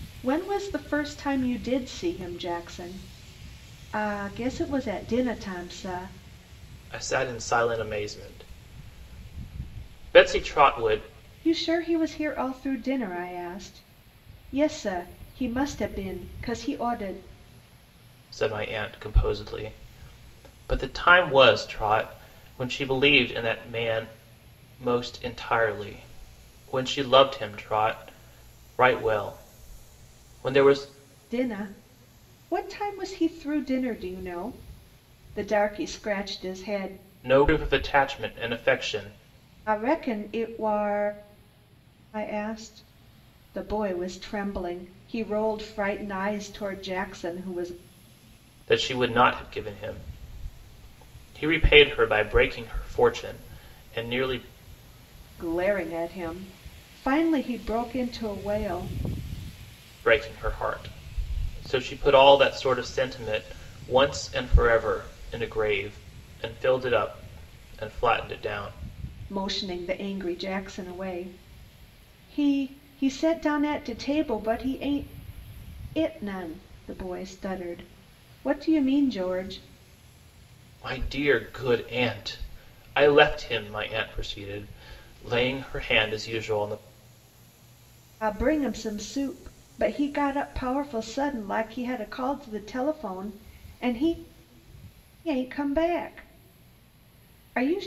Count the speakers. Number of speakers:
two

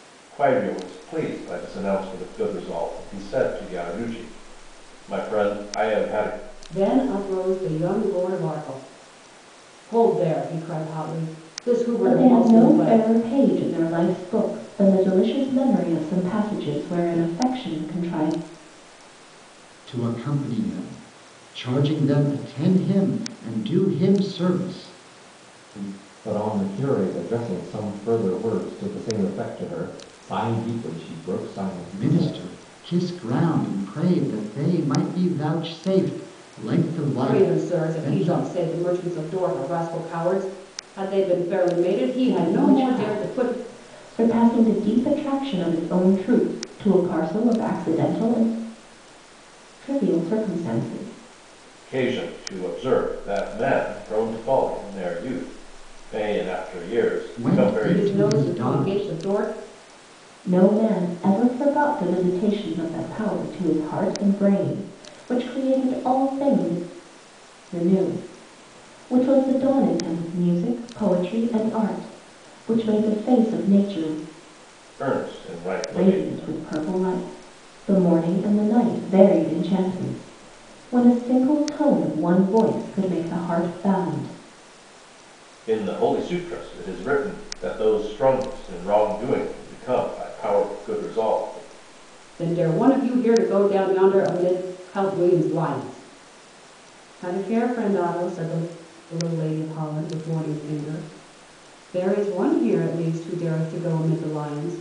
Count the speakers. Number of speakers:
five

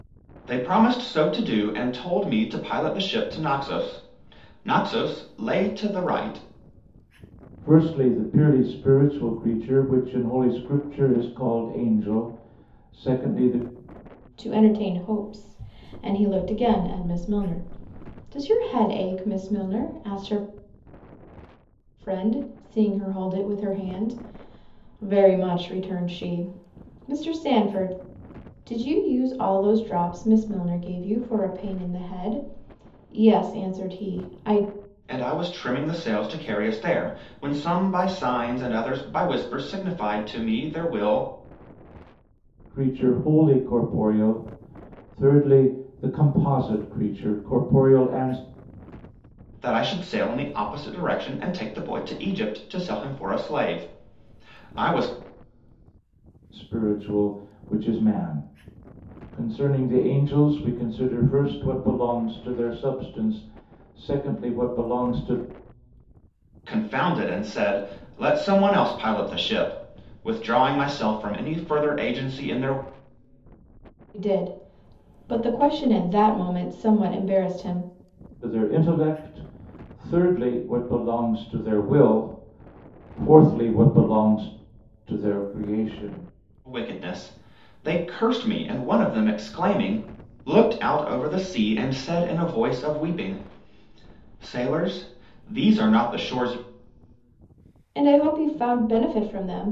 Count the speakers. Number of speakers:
three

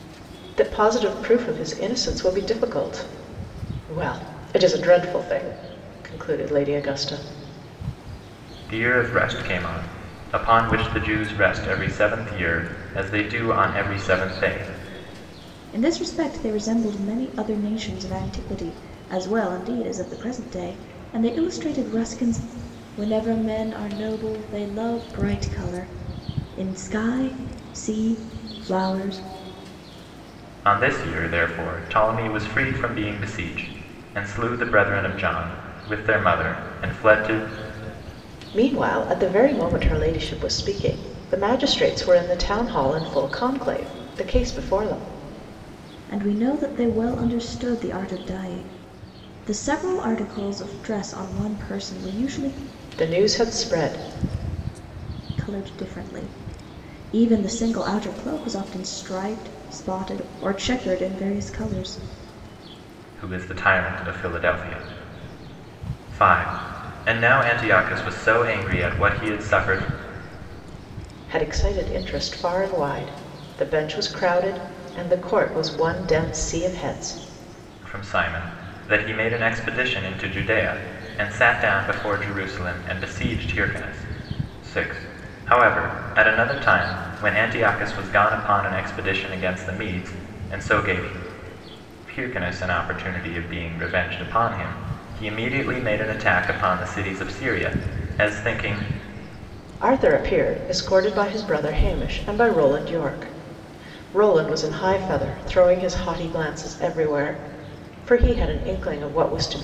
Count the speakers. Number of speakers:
three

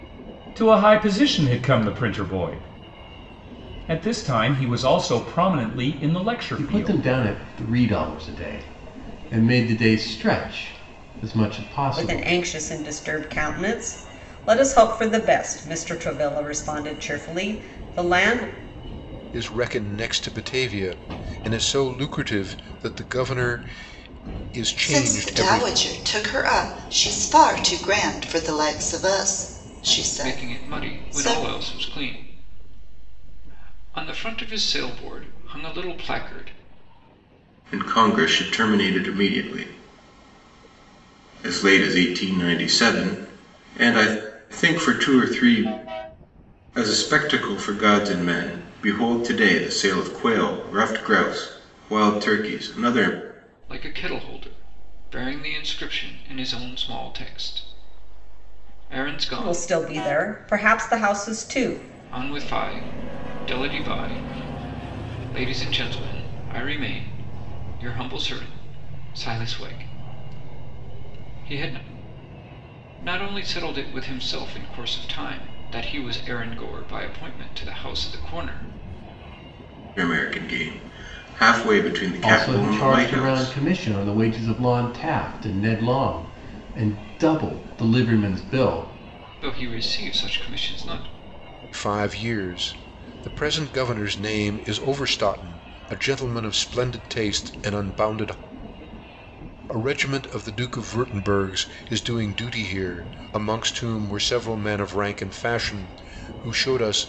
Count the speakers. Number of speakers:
seven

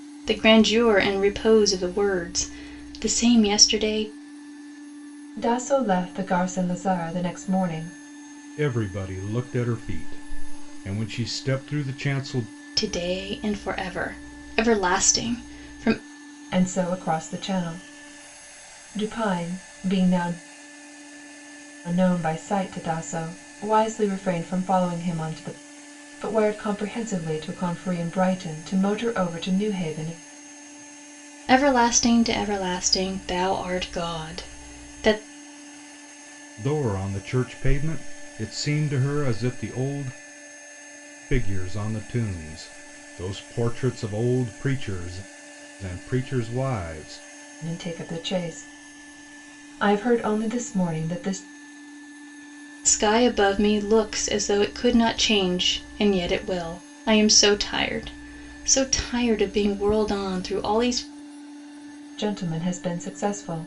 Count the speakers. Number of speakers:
three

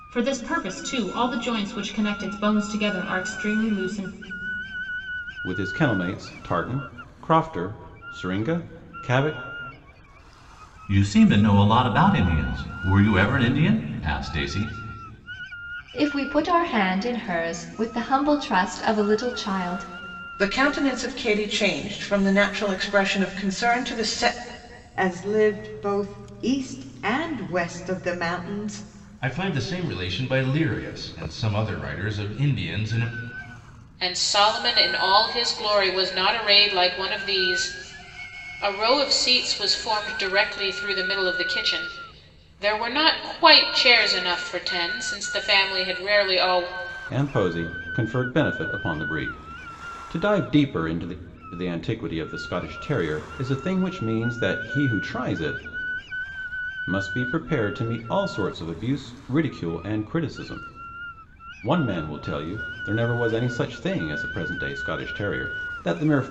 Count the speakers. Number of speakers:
eight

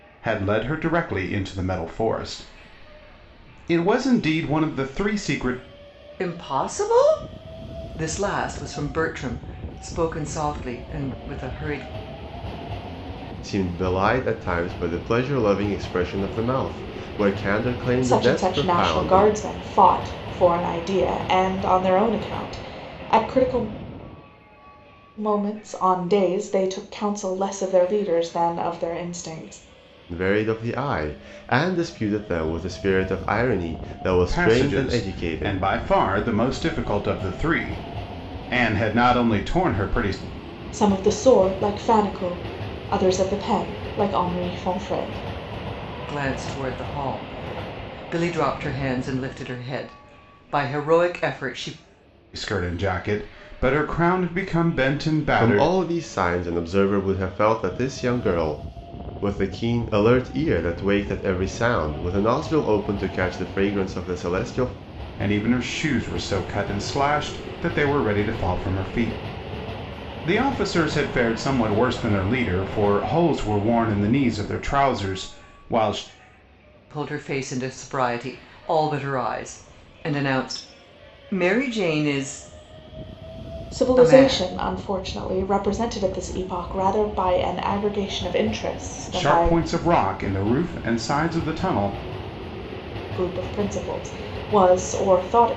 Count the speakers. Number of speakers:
four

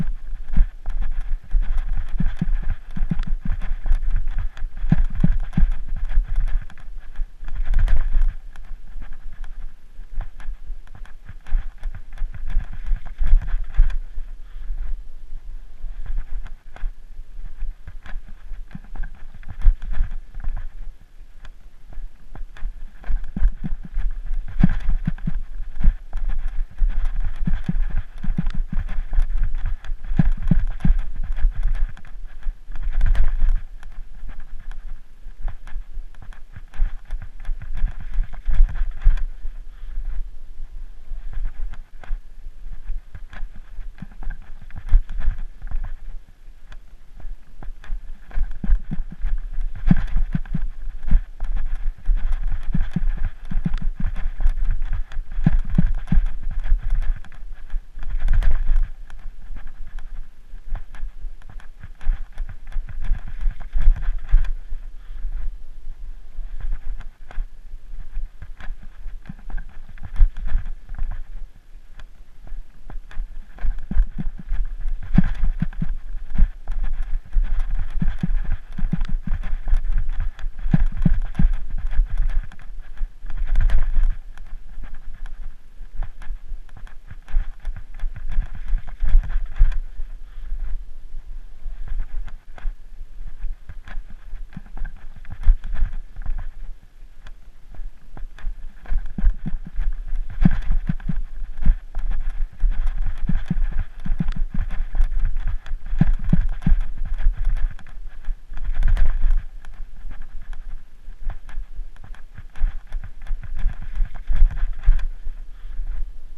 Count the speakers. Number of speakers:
zero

